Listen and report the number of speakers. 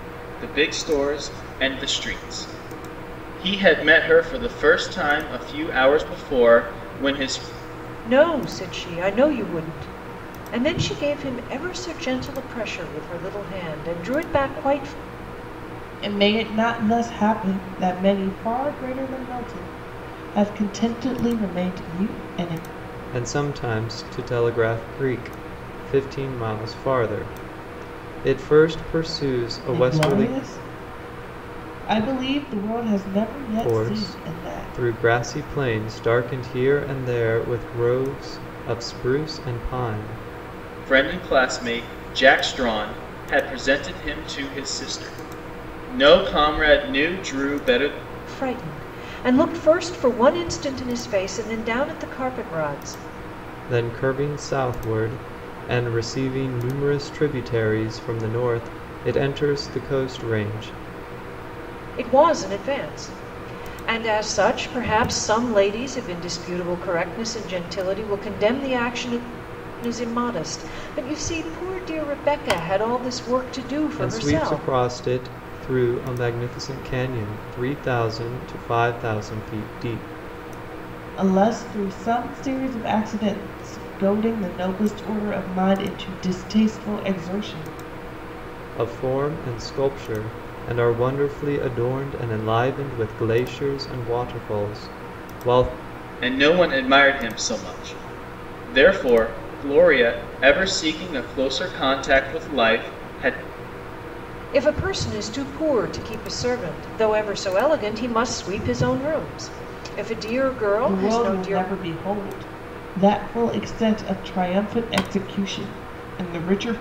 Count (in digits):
4